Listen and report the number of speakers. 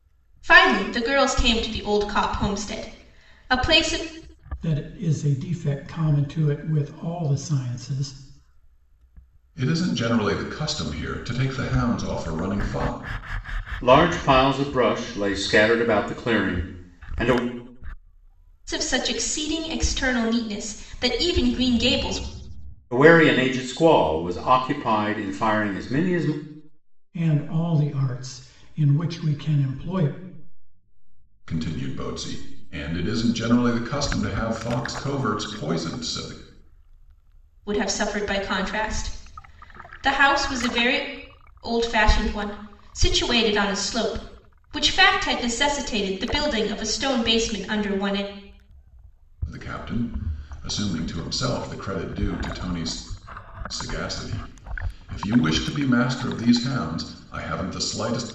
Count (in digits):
4